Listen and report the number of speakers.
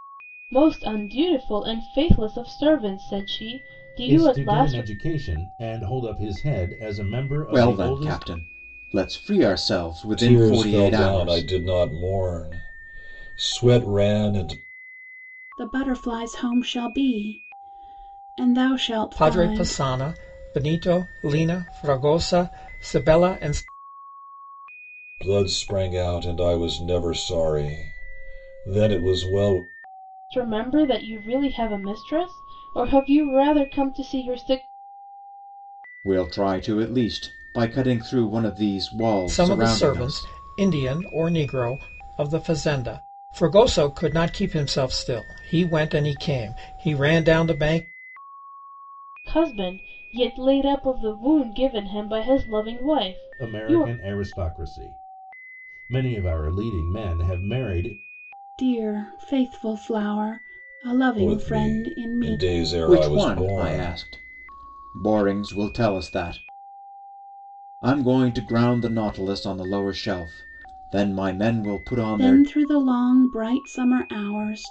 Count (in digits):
6